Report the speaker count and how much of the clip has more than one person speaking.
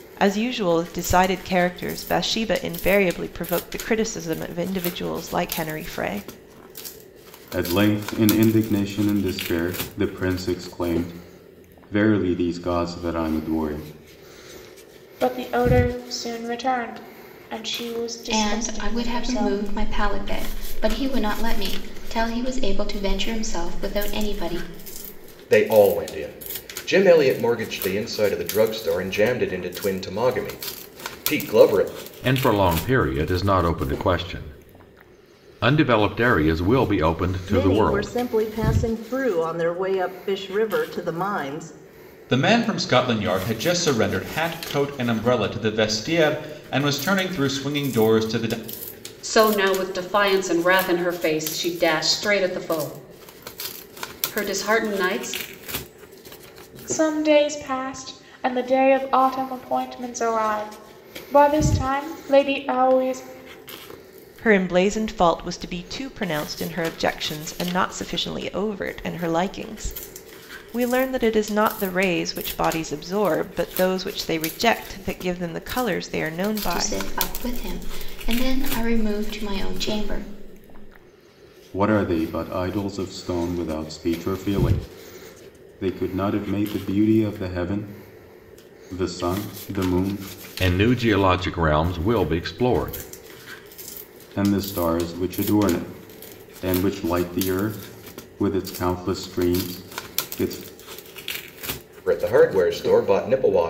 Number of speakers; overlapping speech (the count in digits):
9, about 2%